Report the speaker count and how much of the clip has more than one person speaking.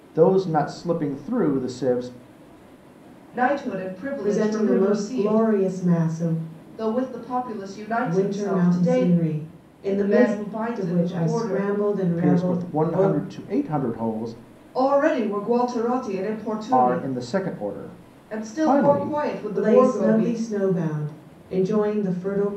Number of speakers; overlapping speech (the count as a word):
three, about 31%